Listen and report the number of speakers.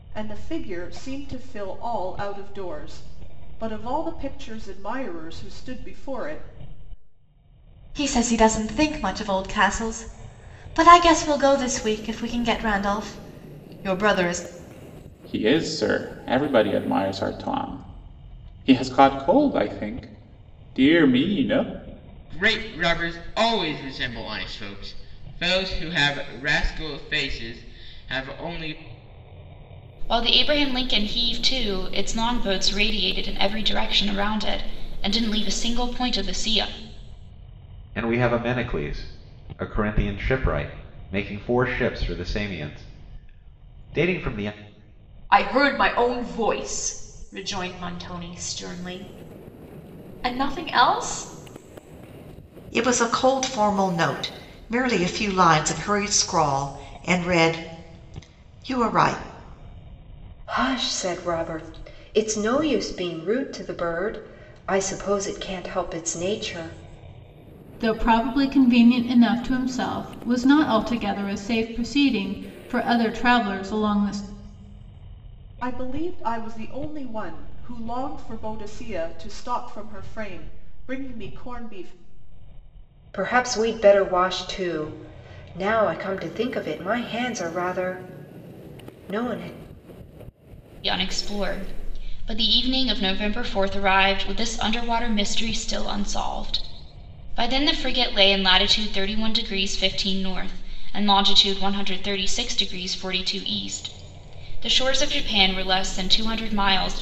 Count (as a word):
ten